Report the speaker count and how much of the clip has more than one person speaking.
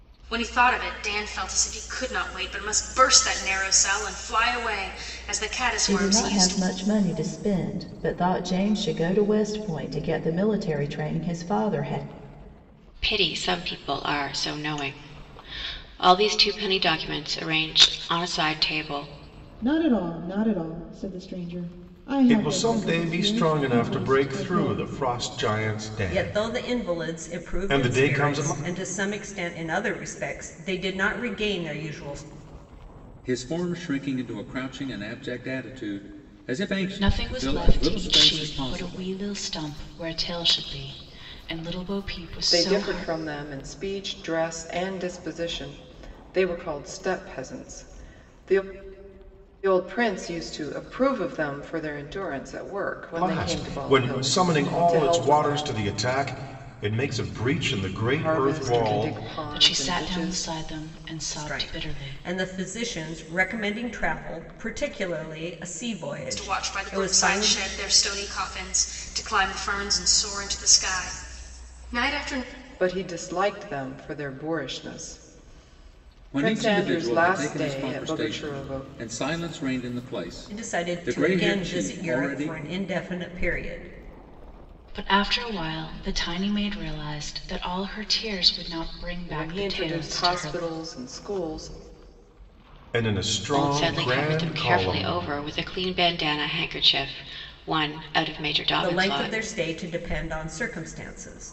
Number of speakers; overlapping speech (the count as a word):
nine, about 24%